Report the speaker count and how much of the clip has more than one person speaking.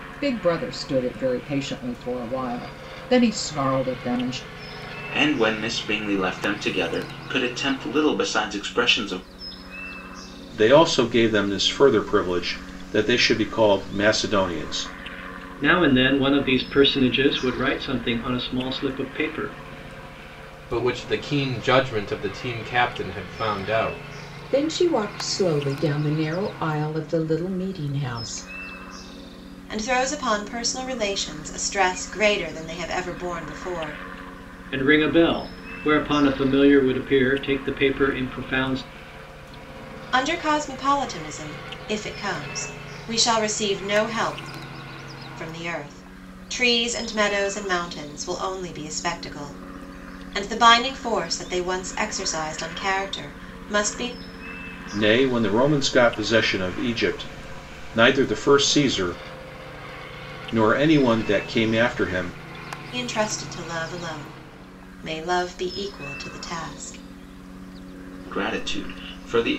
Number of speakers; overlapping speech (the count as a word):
seven, no overlap